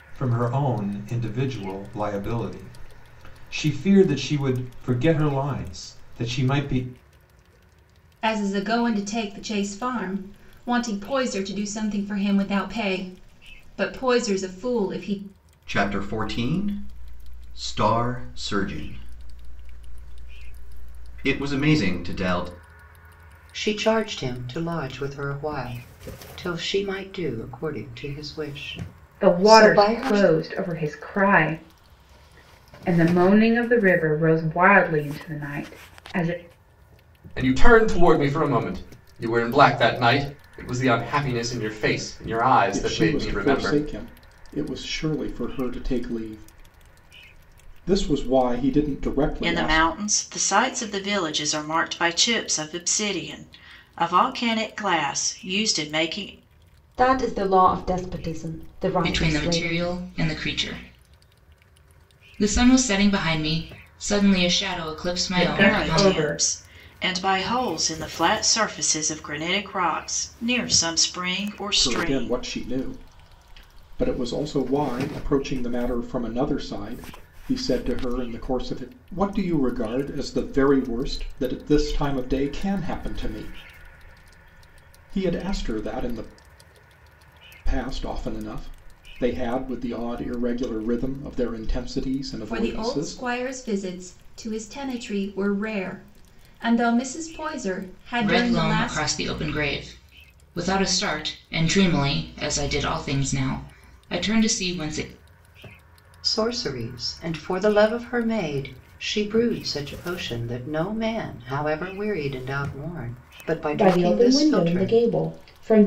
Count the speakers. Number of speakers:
10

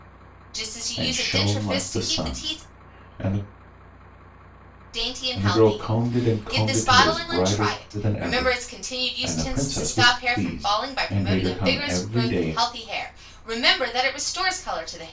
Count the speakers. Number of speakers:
2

